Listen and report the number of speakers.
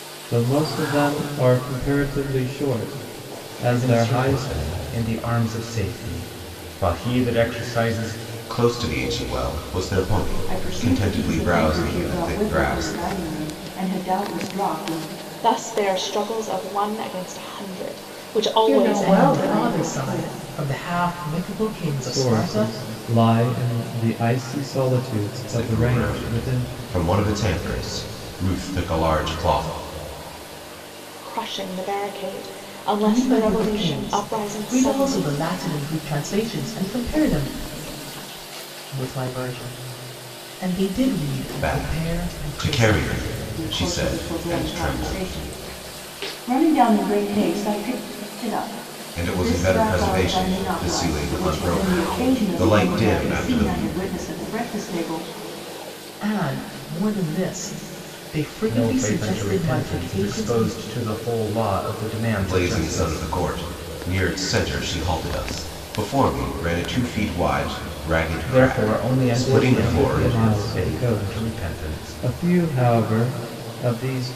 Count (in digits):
7